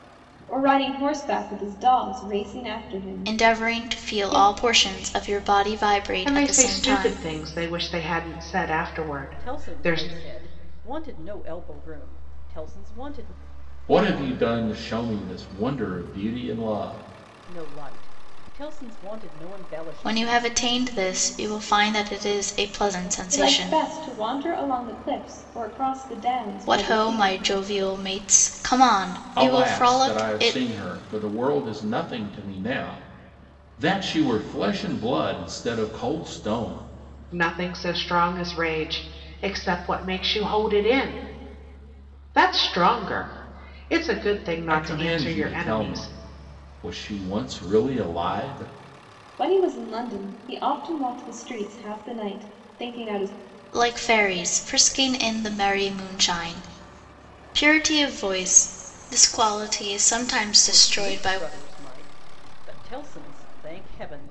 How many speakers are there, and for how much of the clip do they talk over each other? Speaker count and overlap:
five, about 13%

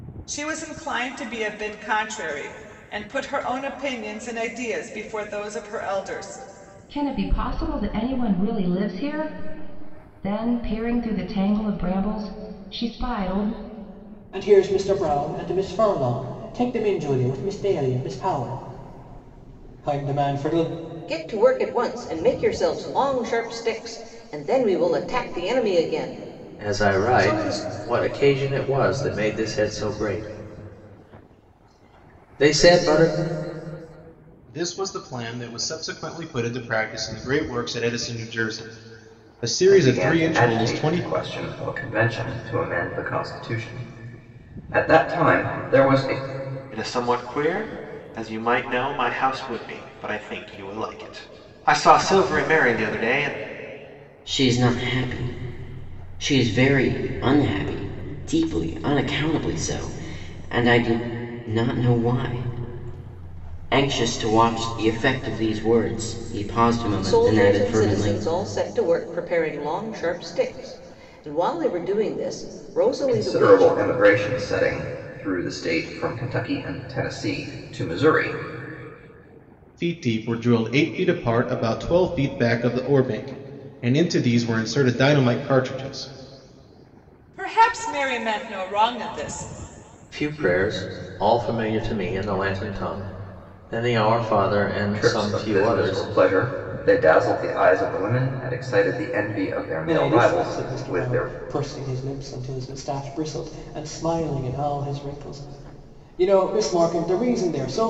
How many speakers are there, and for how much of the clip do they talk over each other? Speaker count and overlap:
nine, about 7%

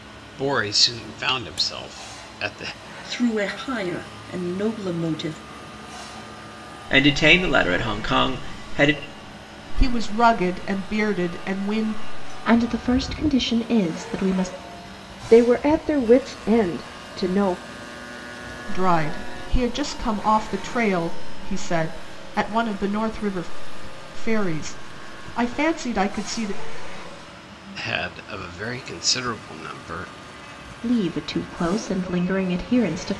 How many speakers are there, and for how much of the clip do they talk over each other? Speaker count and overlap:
six, no overlap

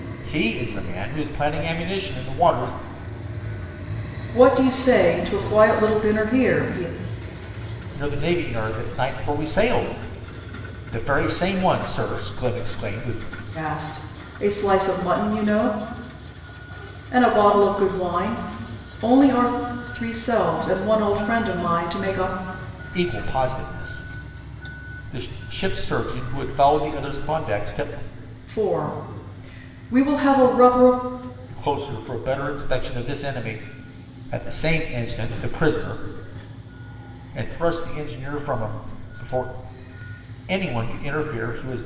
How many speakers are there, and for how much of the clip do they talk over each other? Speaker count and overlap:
two, no overlap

